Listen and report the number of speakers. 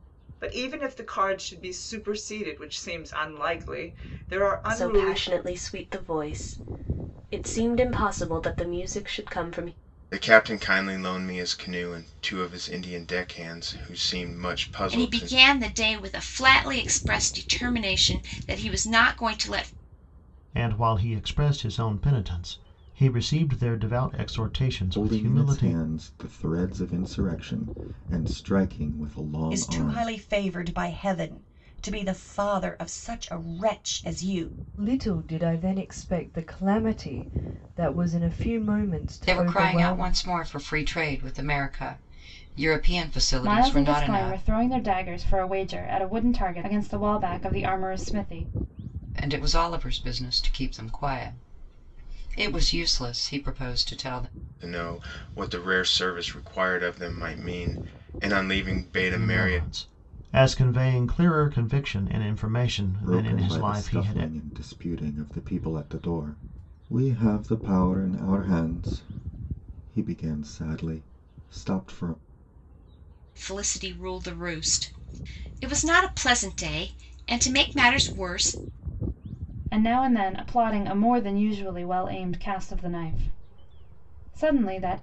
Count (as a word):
ten